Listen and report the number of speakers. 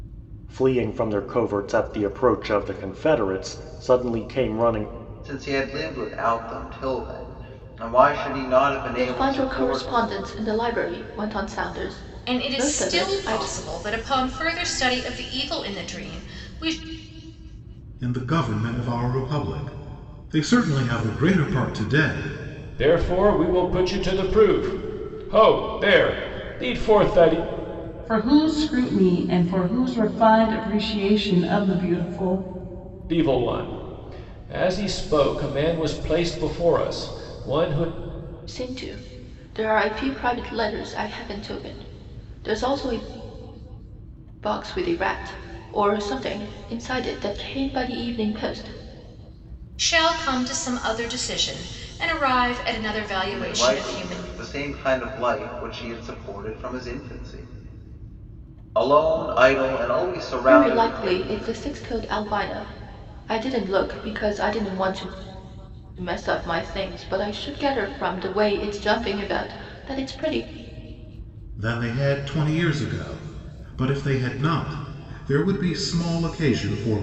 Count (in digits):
7